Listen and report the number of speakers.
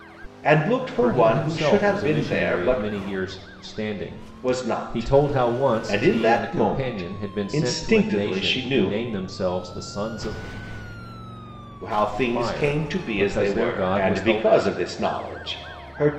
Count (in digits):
2